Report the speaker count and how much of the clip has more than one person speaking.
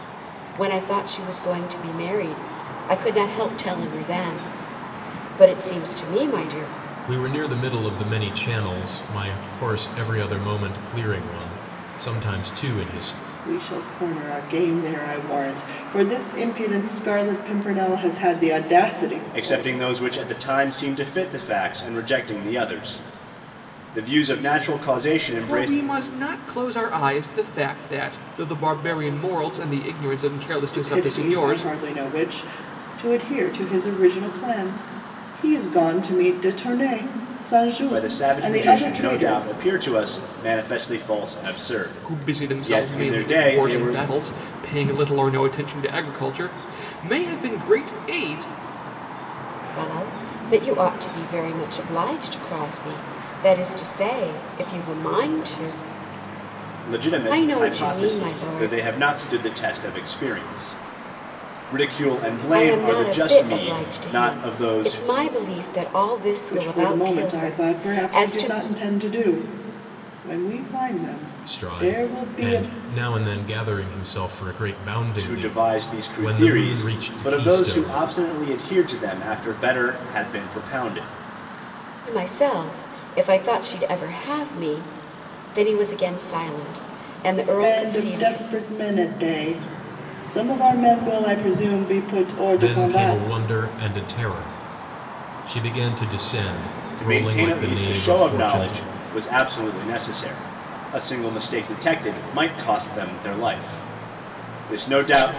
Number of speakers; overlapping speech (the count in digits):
5, about 19%